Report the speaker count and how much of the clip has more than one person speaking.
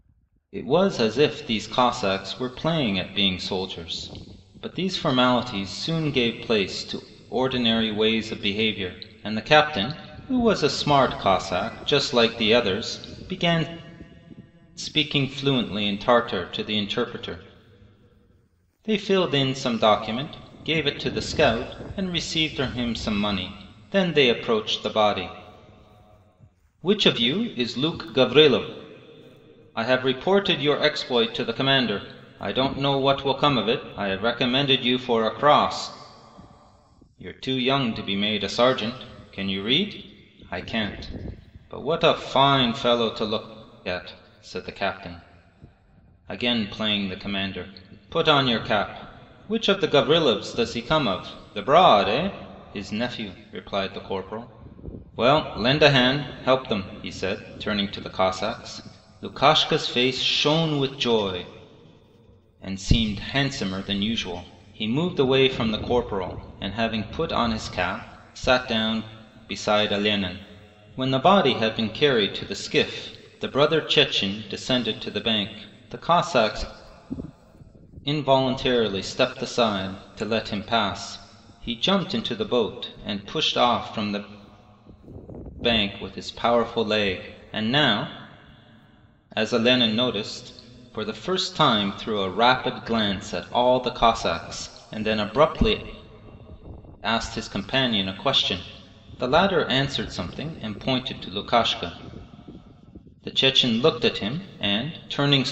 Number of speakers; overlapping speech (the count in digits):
1, no overlap